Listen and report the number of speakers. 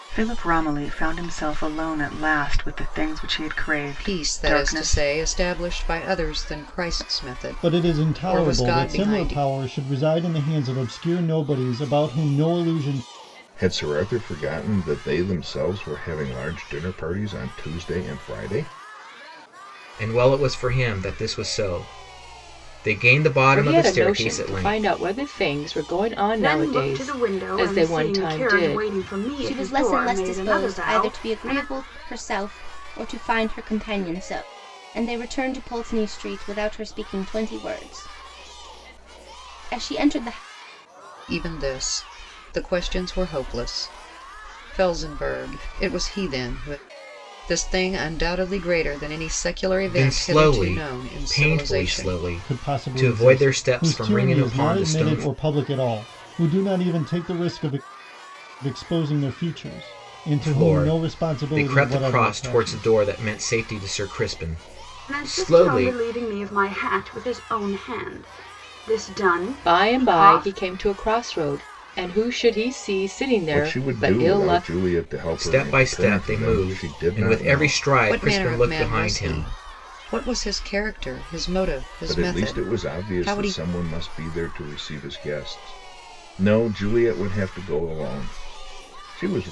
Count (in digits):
8